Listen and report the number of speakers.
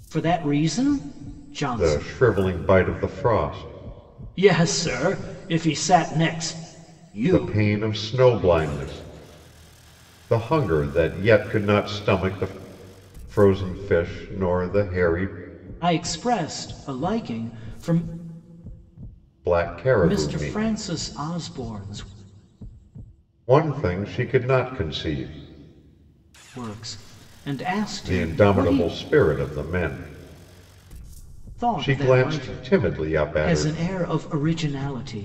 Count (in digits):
2